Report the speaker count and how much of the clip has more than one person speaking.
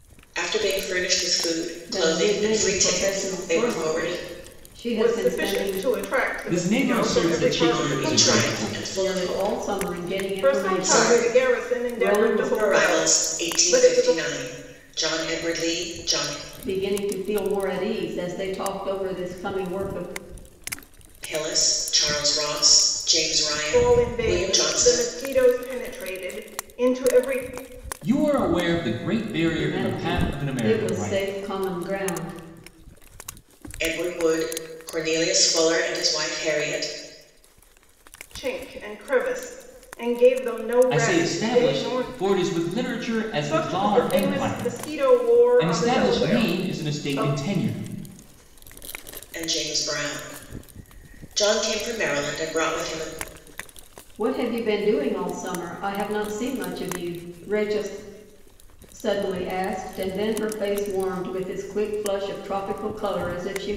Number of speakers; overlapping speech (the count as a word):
four, about 29%